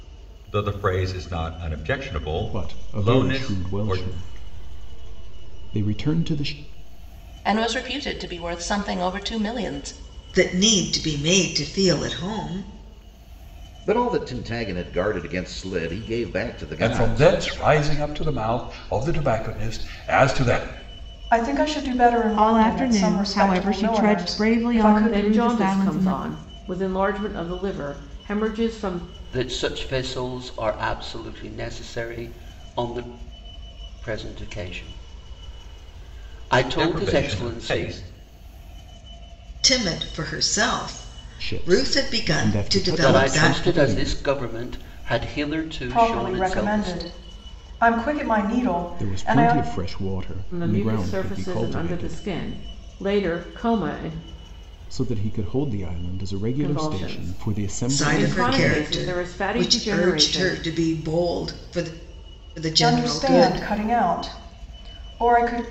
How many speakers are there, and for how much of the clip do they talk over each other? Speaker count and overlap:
10, about 28%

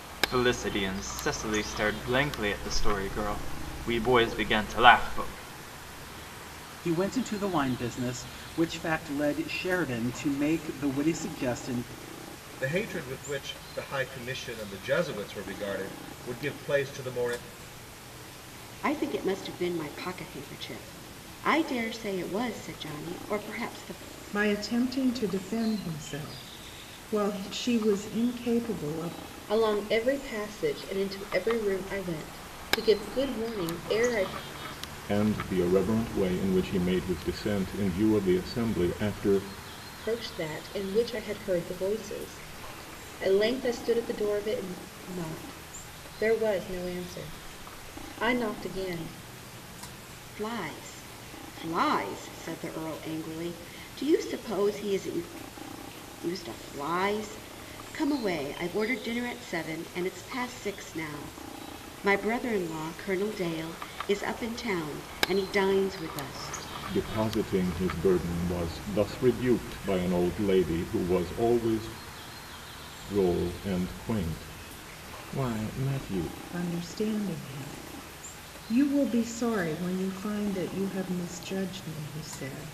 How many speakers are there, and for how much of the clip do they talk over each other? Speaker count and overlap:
7, no overlap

